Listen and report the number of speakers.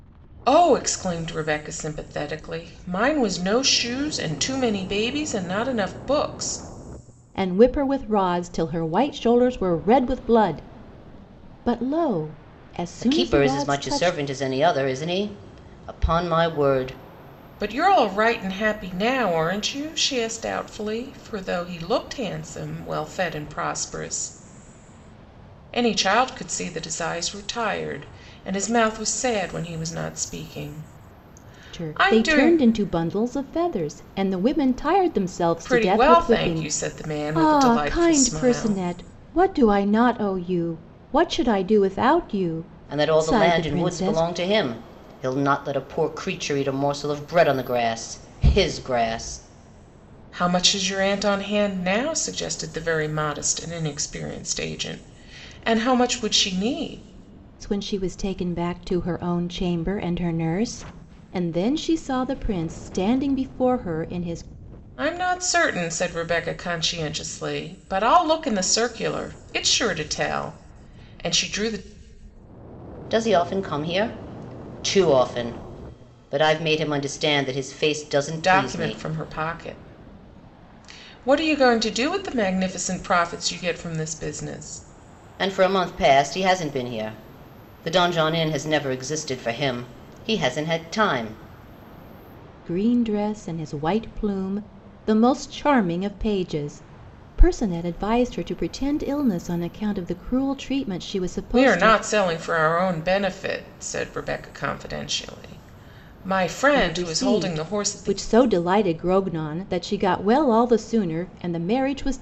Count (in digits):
3